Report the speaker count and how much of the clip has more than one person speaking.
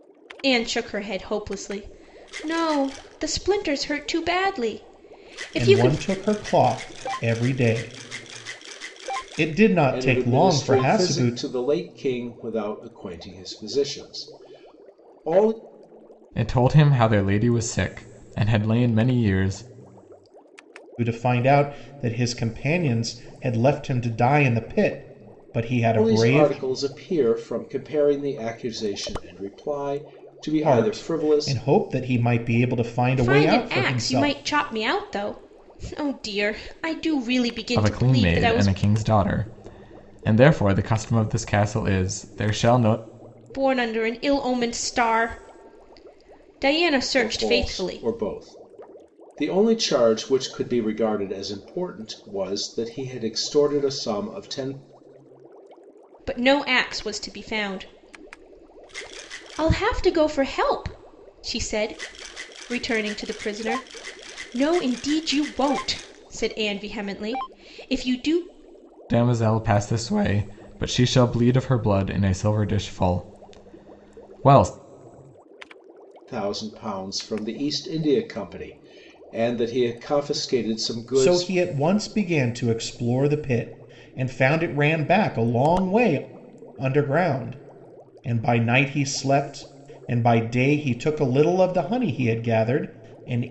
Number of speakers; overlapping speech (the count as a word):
four, about 8%